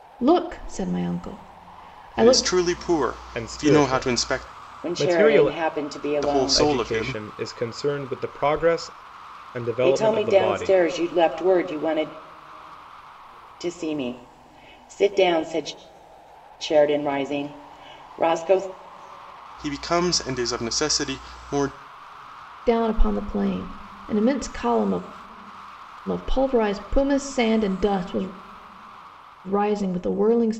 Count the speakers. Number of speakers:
four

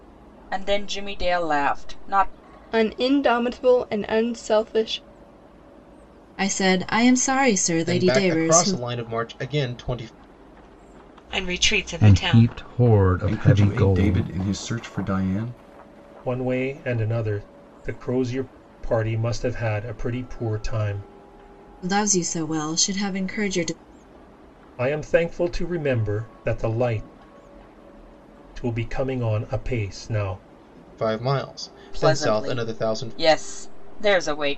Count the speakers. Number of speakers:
eight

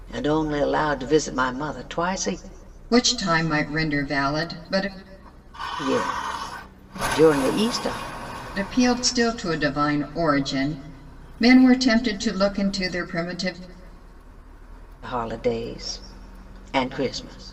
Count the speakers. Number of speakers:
two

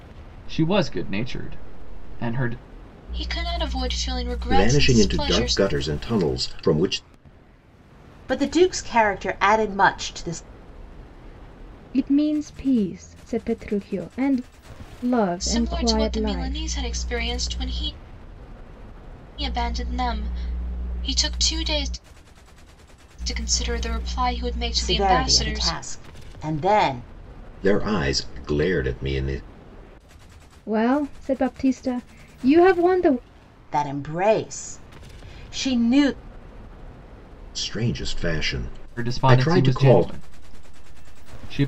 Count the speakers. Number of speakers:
five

